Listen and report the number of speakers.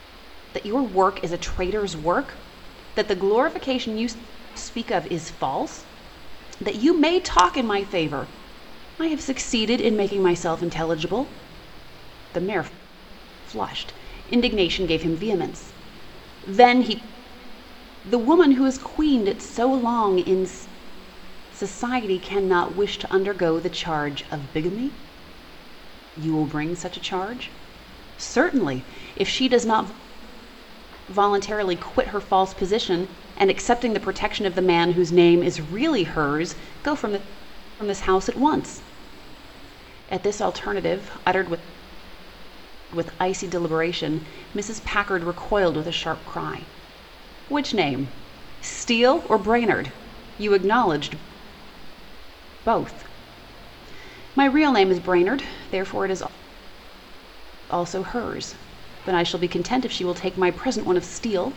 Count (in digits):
1